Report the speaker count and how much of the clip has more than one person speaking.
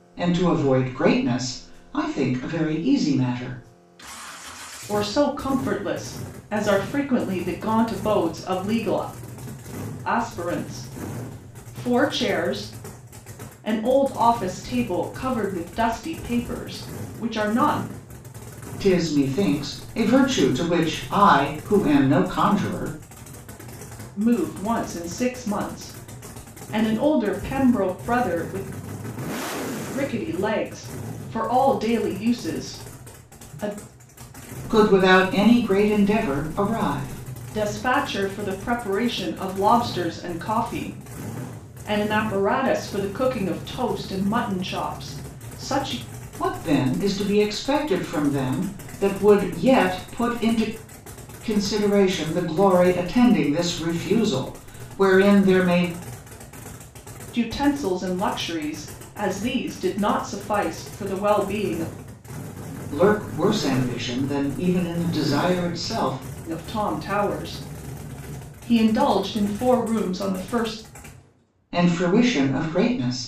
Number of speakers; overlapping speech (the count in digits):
2, no overlap